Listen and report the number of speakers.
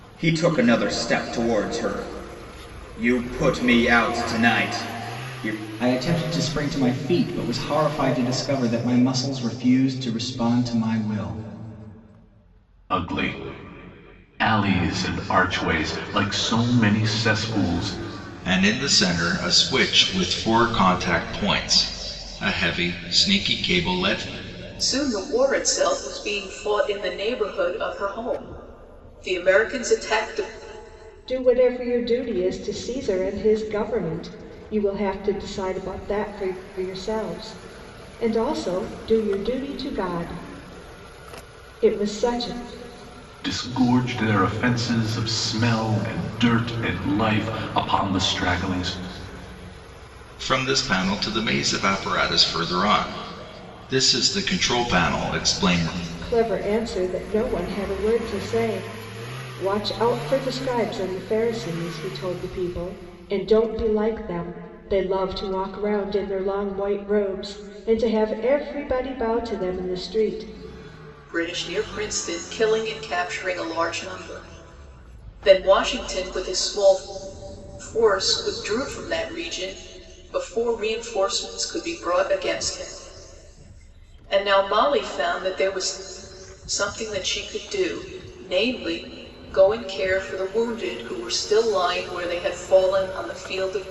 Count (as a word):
six